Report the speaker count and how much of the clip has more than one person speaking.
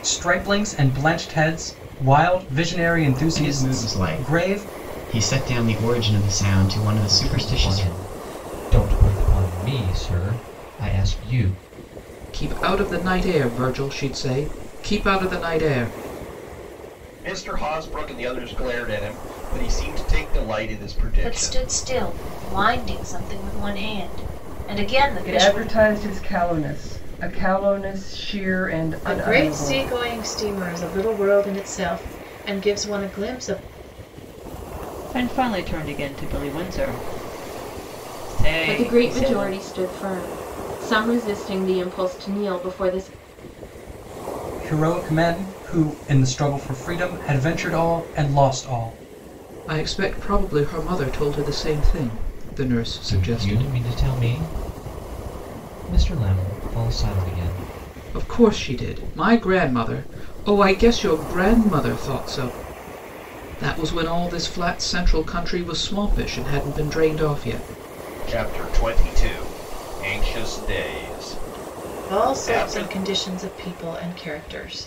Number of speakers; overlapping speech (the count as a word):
ten, about 9%